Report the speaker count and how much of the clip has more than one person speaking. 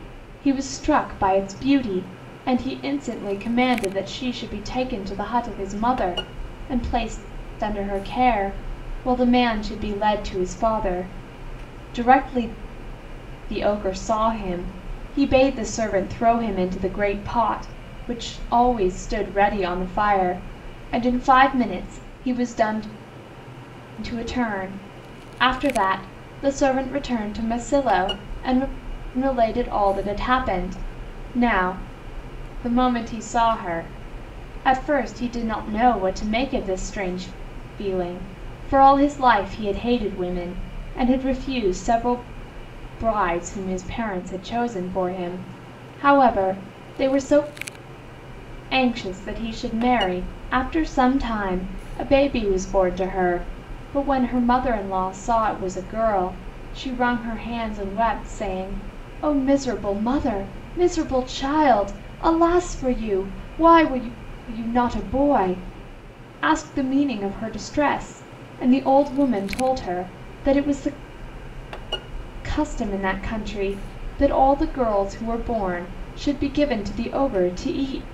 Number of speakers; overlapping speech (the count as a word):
one, no overlap